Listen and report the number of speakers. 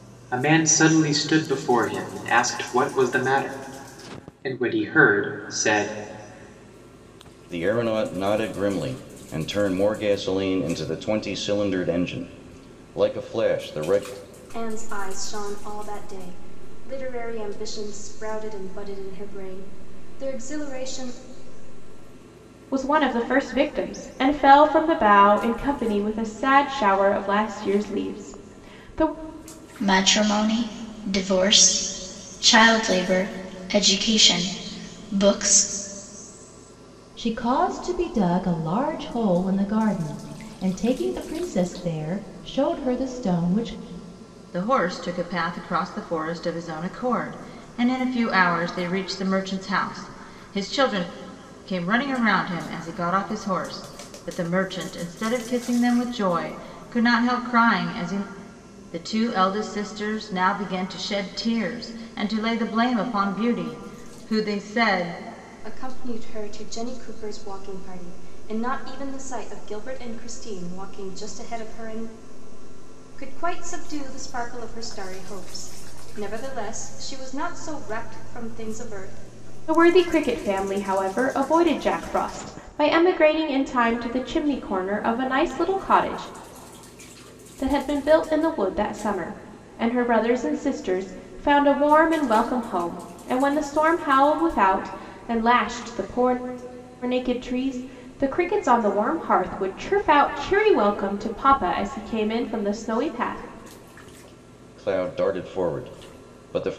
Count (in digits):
7